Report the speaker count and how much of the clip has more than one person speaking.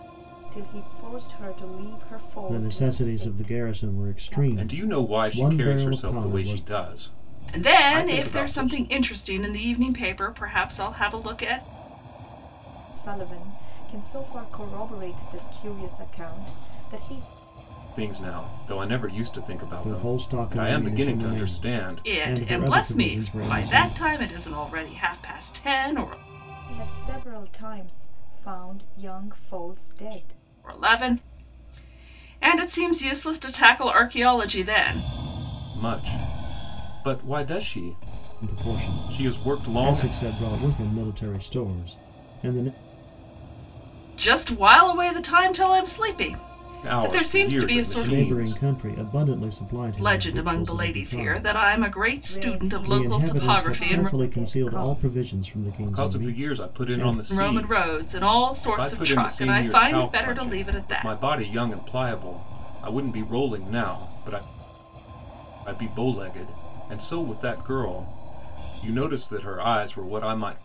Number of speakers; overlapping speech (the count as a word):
four, about 33%